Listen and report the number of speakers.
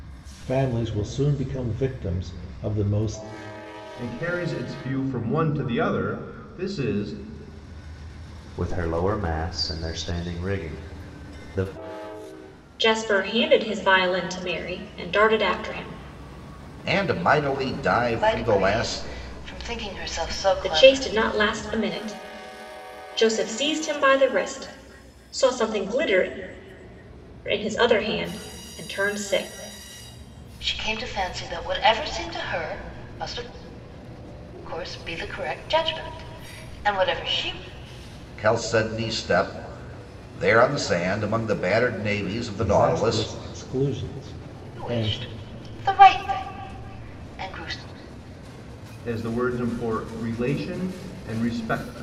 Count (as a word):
six